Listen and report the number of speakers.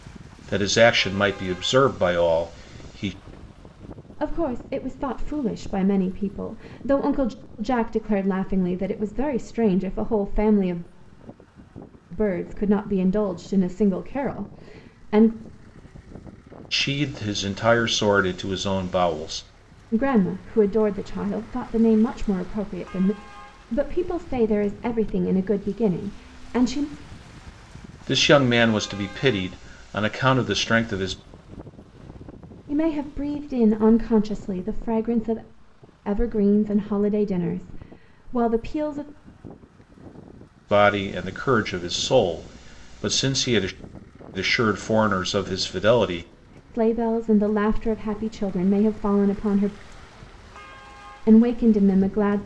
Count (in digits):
2